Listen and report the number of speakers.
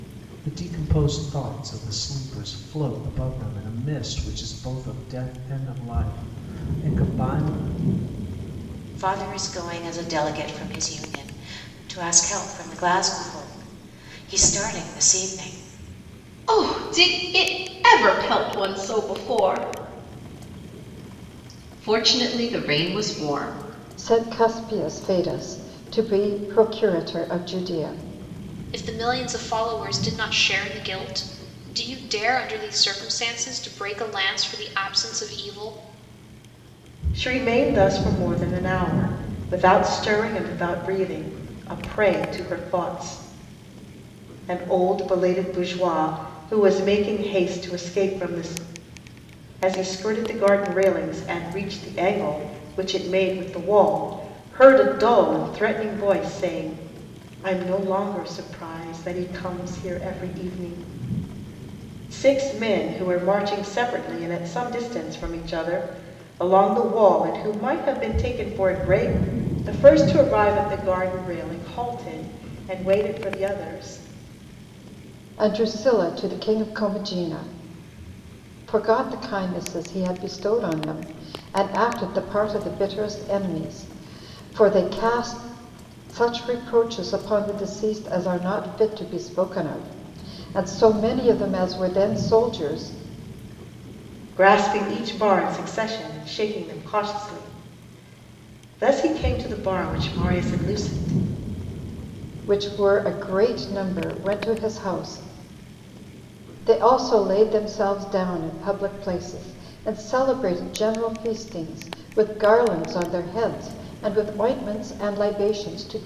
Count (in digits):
6